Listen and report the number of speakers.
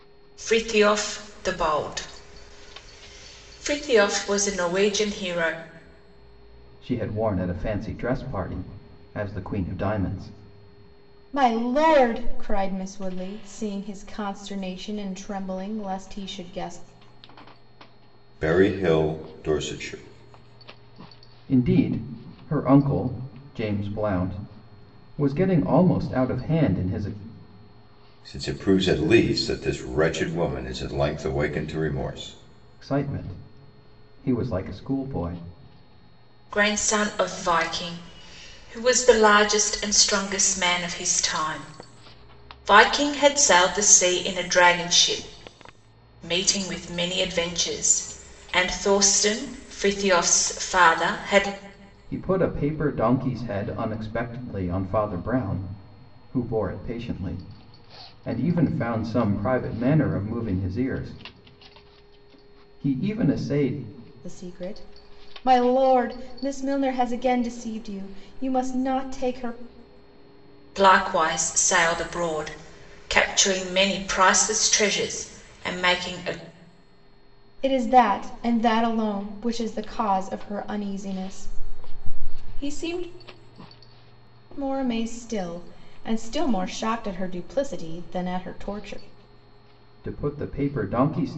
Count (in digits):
4